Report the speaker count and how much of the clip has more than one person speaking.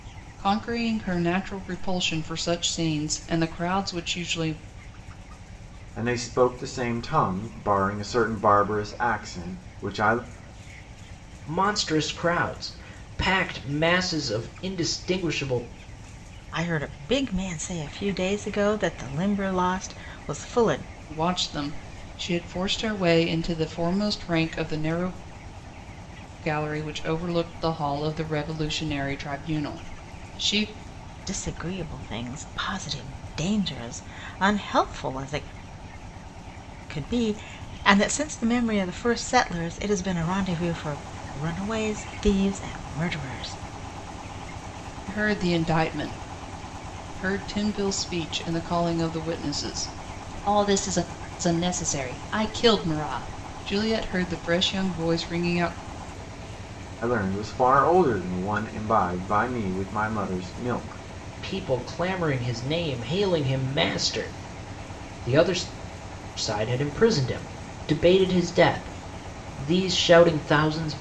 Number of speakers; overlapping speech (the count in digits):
4, no overlap